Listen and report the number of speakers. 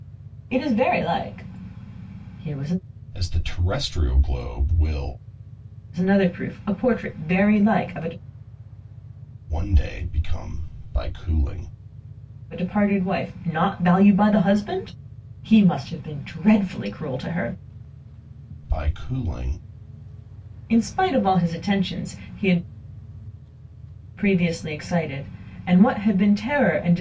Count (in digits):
2